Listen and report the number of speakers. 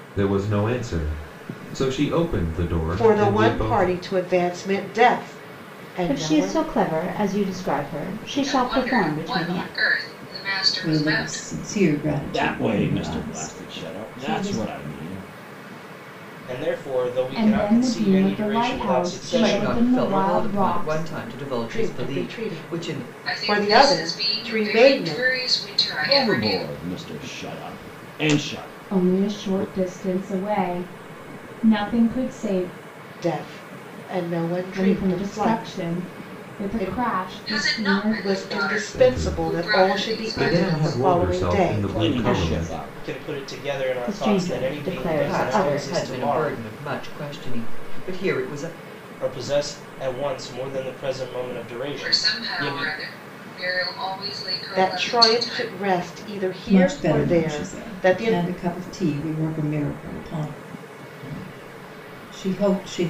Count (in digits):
9